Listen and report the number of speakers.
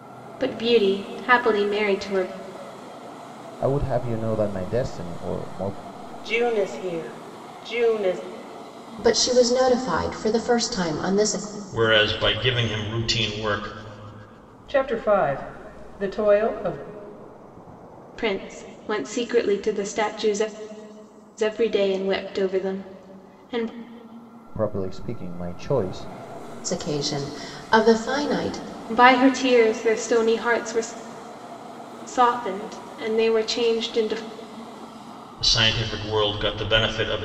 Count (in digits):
6